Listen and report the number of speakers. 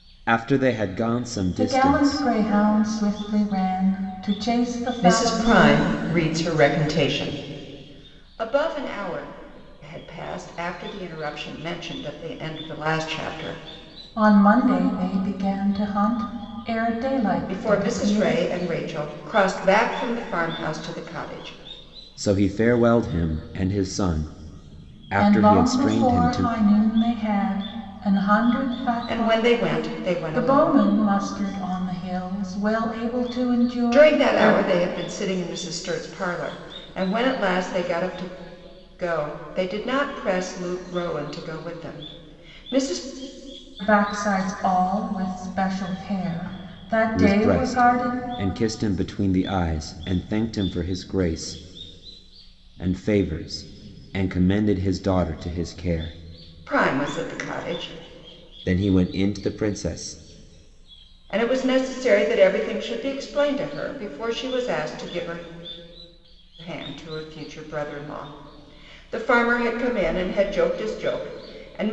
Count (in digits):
3